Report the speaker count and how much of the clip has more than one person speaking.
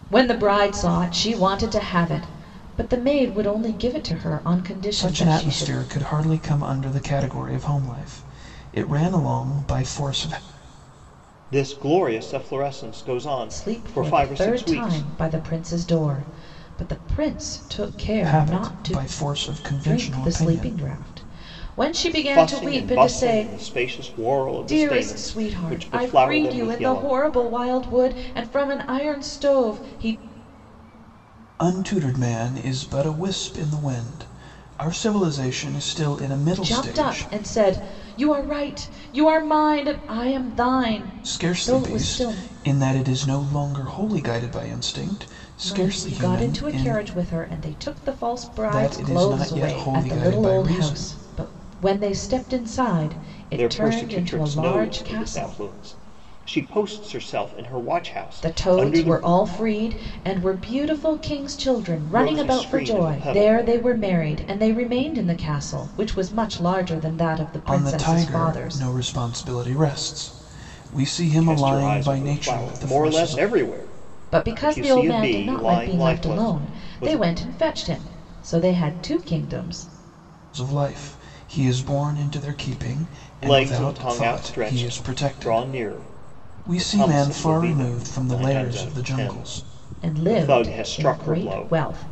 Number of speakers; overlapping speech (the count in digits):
3, about 34%